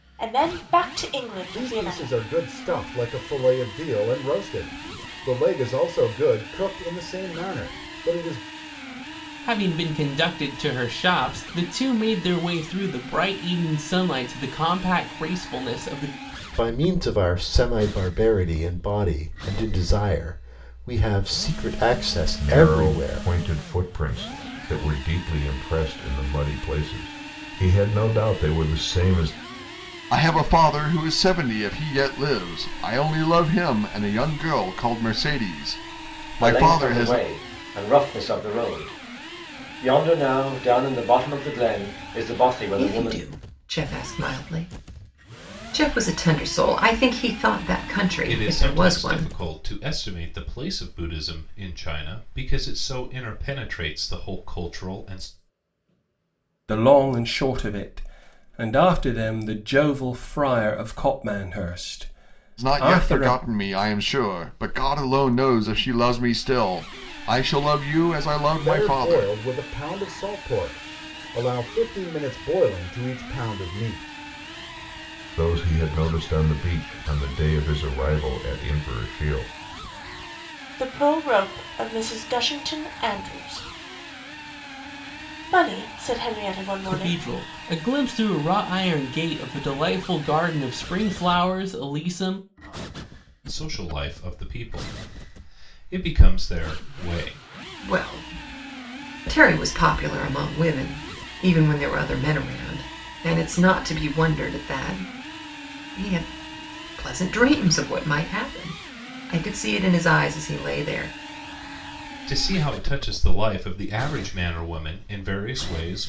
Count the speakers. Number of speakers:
10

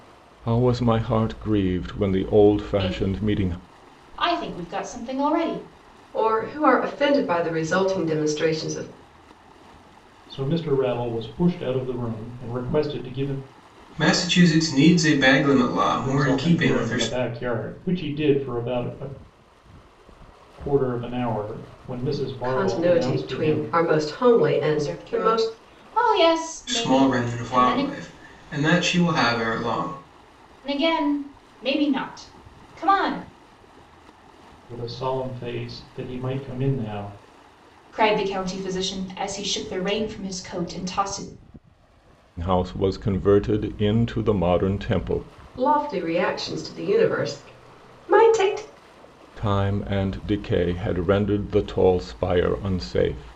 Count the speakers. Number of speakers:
5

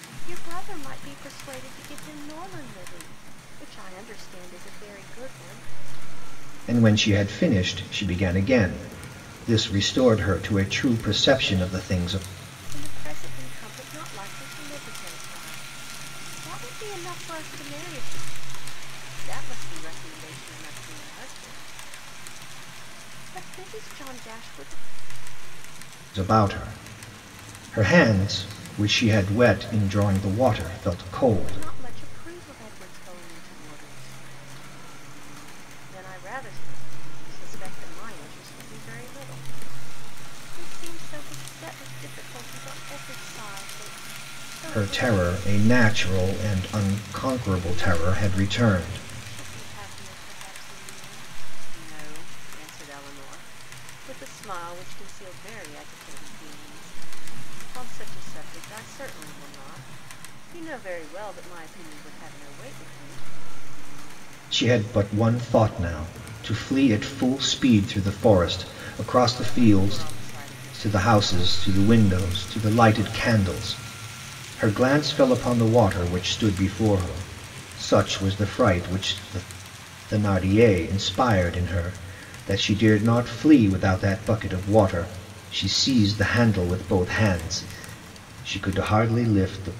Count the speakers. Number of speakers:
2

